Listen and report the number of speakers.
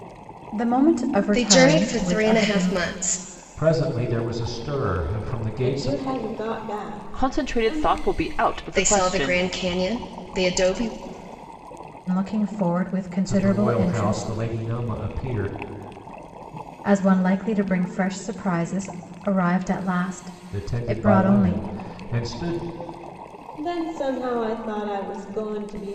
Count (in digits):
5